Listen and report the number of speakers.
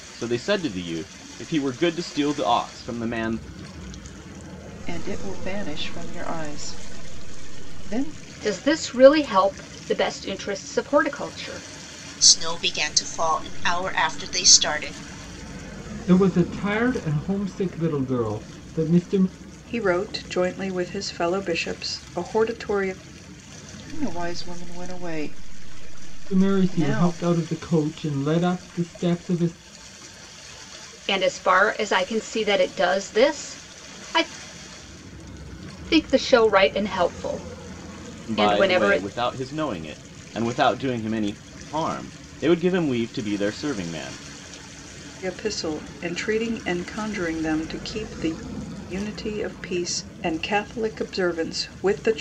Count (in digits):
6